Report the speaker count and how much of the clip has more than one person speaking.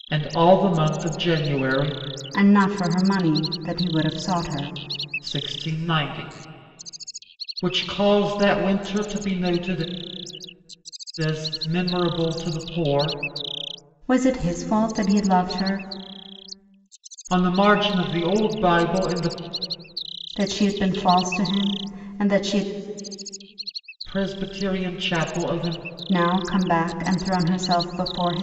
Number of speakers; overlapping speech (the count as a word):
two, no overlap